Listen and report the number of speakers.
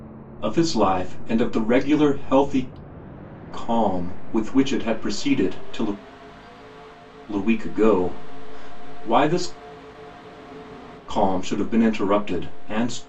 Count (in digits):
1